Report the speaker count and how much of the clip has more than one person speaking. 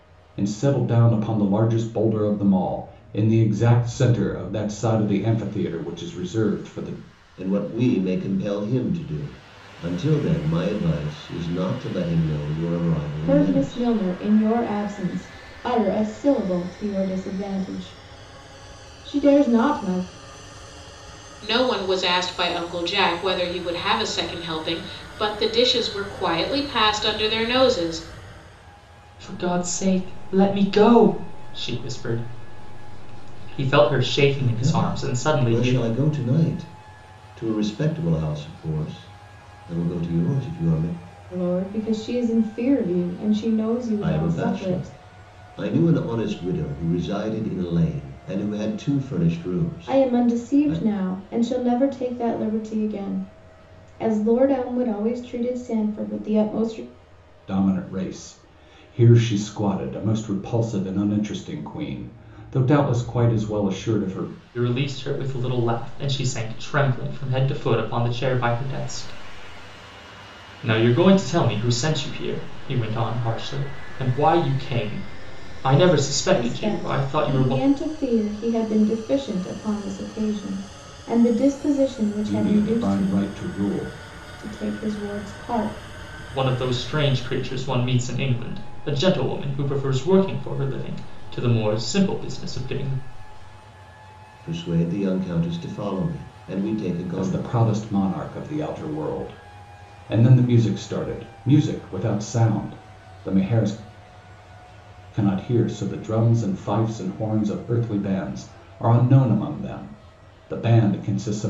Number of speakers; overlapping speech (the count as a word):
five, about 6%